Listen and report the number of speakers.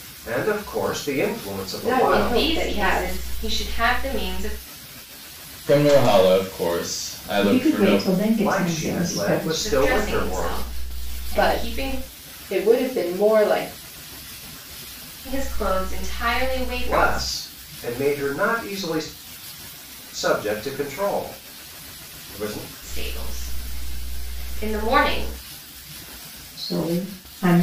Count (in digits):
5